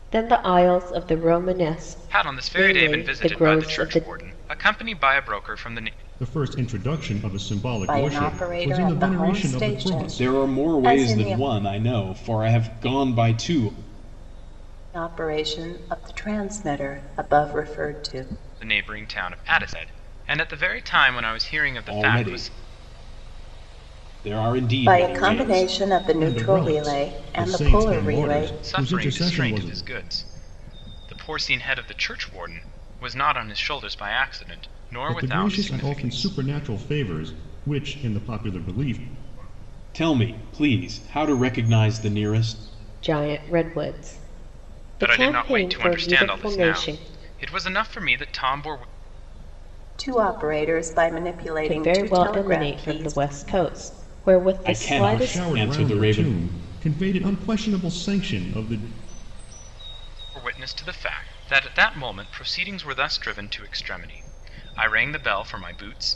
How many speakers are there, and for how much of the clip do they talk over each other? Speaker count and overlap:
5, about 26%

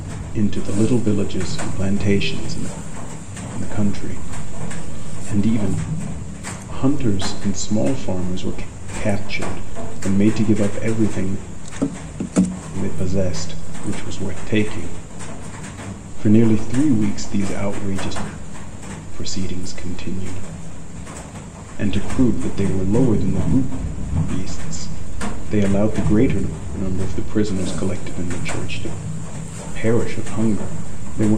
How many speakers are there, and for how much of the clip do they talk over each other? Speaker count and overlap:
1, no overlap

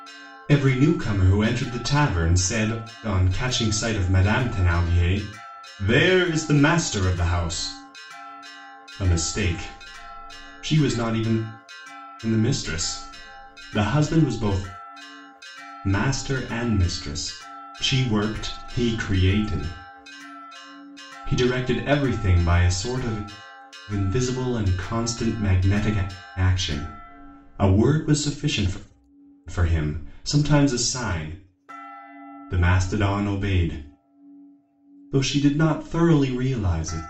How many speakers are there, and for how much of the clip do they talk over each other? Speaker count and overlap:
1, no overlap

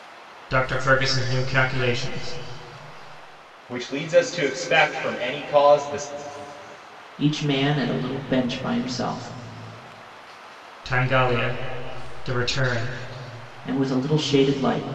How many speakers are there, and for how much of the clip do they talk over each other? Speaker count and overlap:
3, no overlap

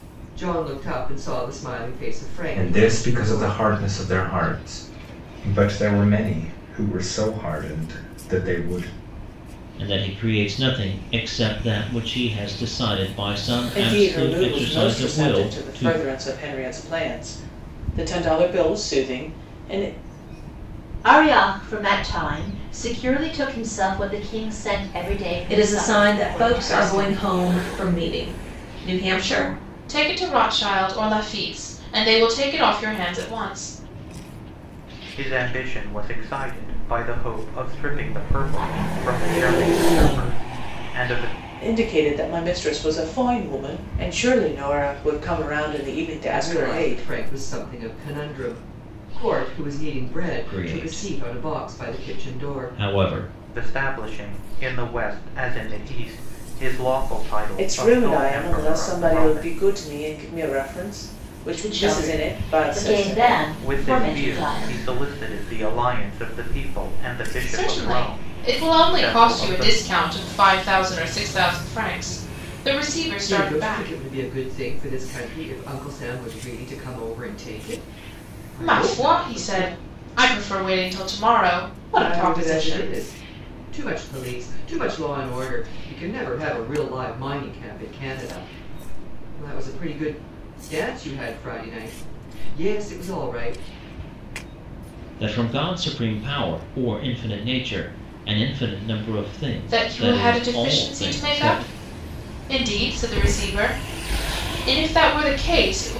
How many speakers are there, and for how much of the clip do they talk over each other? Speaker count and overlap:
8, about 20%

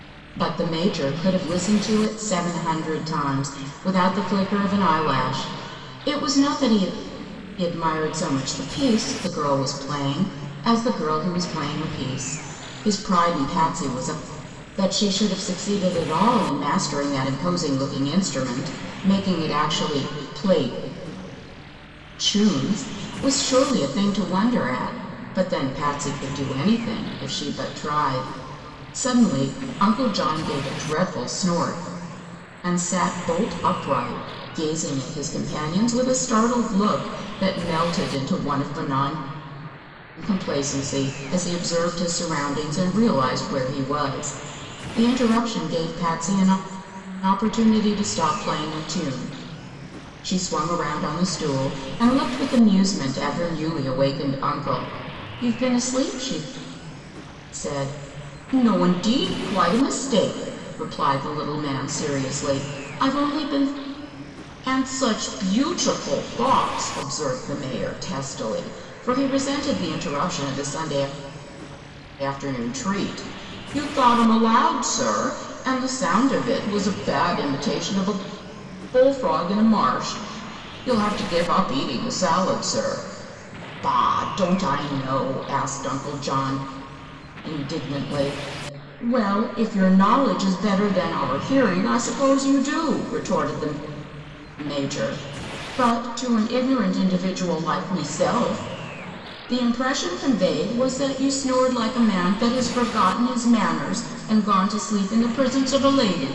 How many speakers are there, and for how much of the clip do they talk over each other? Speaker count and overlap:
1, no overlap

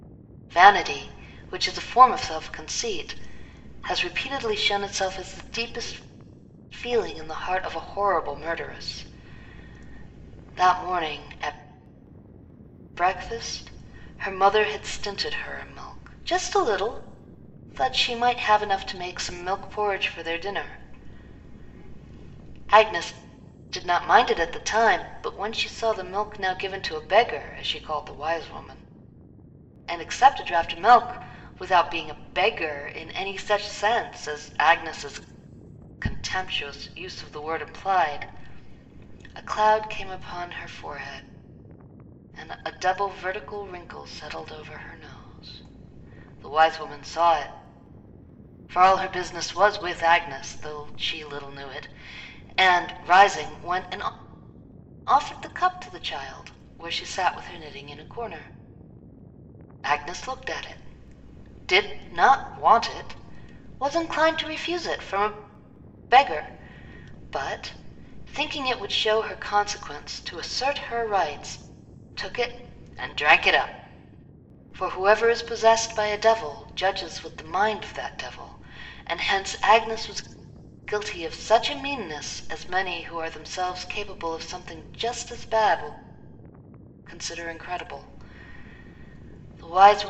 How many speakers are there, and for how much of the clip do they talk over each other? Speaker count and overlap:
1, no overlap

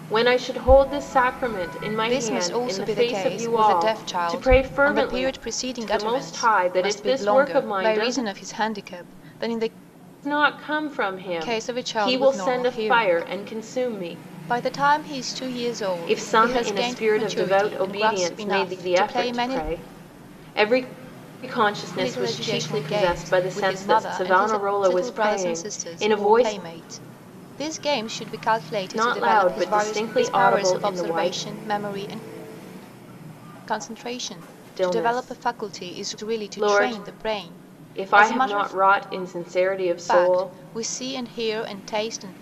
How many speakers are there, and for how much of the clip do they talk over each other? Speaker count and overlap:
2, about 52%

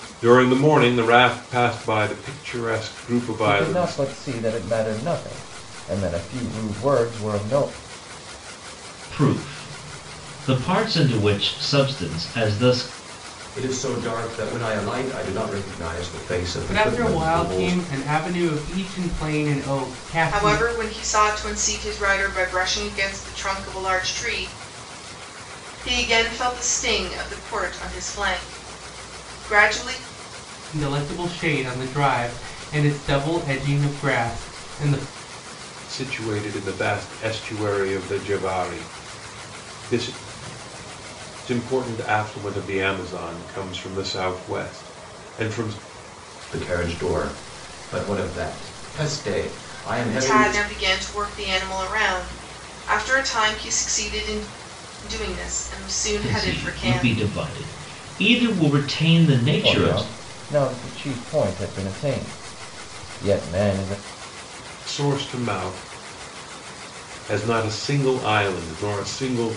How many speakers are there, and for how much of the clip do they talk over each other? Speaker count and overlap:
6, about 6%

